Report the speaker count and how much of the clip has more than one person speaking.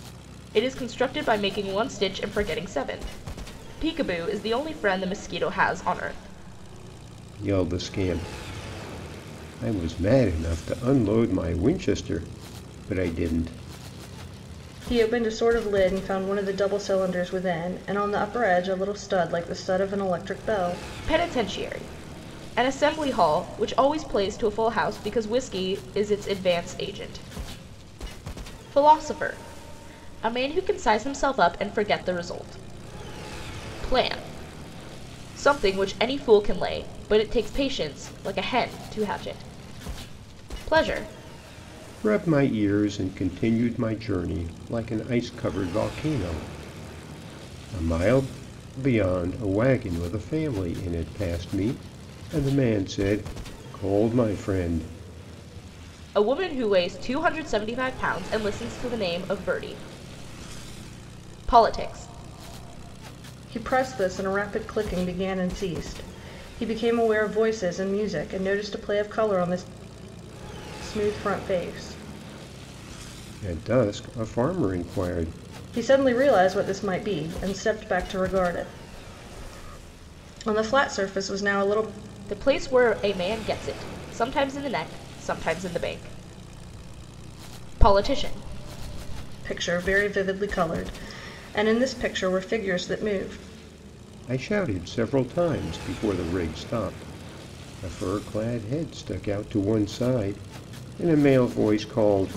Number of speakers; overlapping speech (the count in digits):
3, no overlap